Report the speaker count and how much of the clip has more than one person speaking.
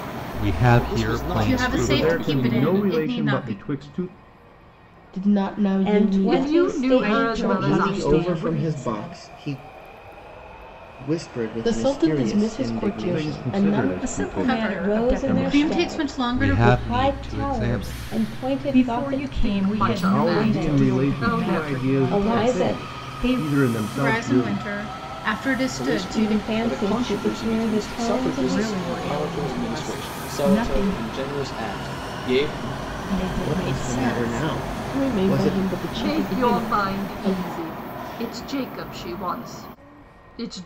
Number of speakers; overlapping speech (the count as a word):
nine, about 66%